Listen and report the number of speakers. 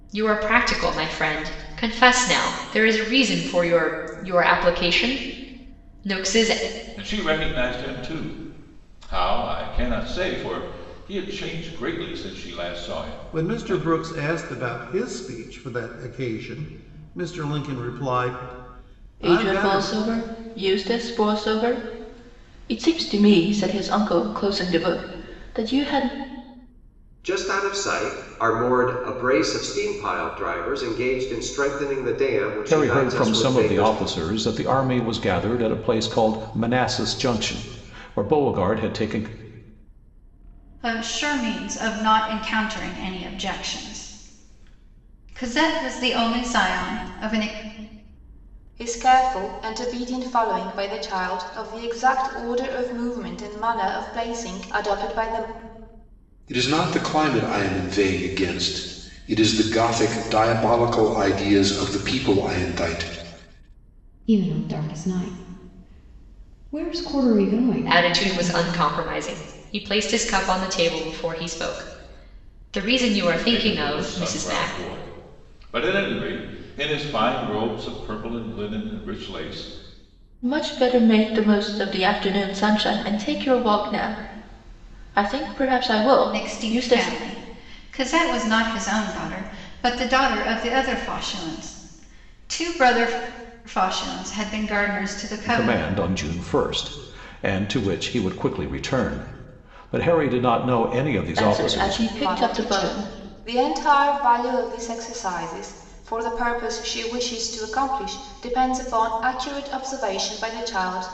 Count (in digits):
10